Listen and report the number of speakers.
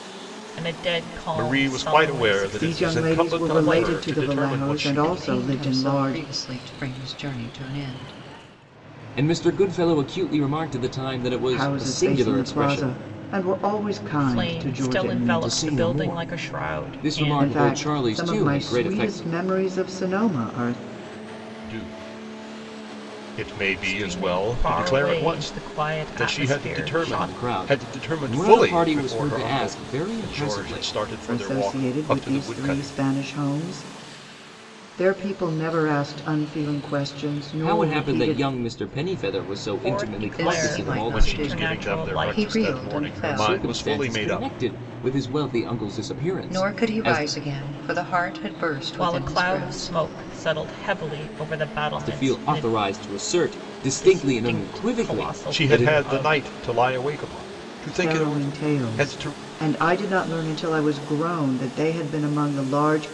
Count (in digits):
5